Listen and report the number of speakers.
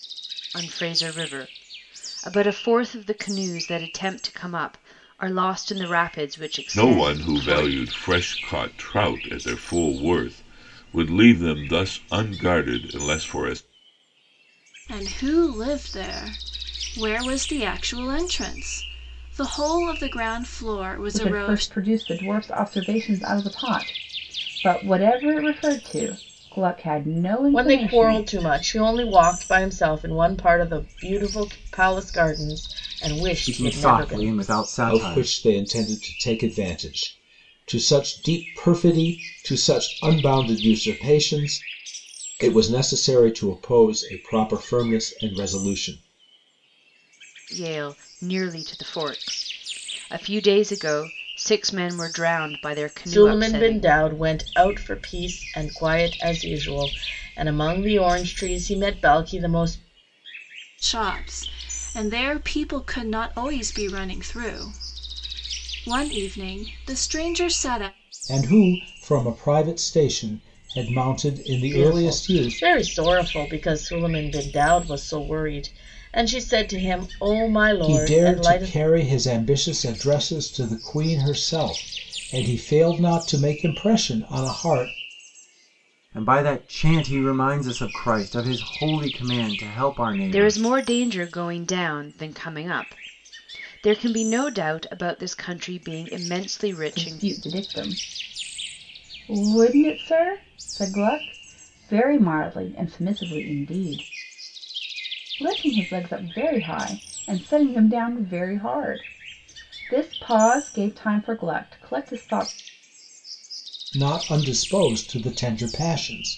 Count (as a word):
seven